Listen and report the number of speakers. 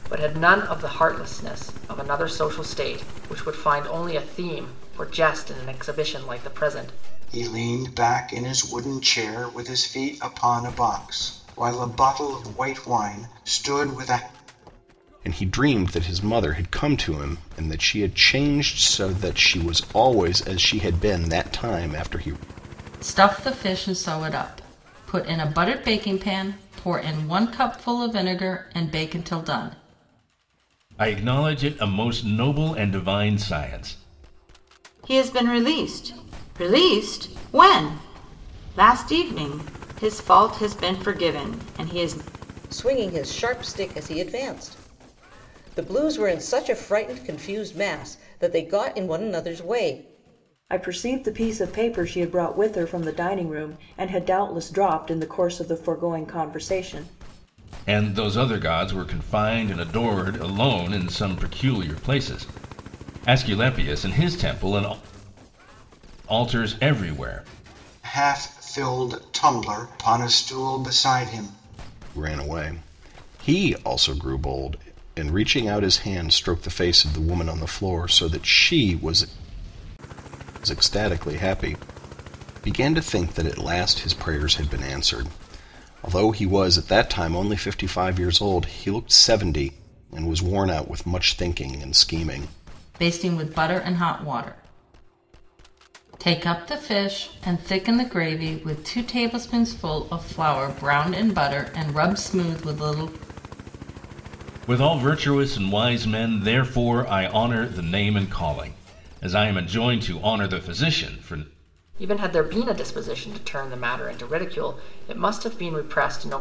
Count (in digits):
8